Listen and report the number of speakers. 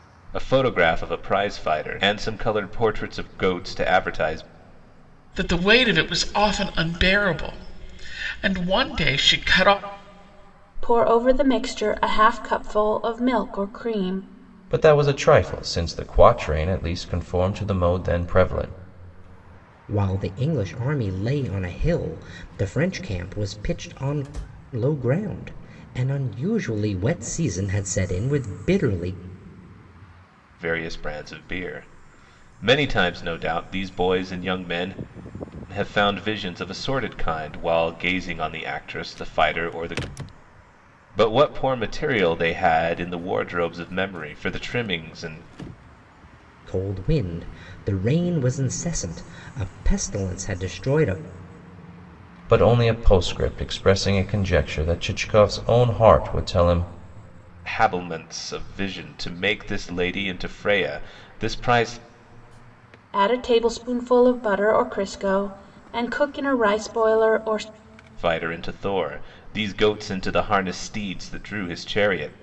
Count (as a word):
five